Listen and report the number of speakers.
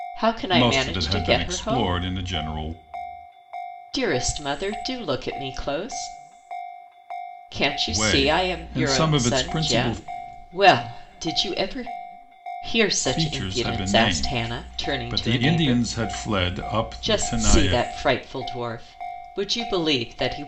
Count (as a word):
two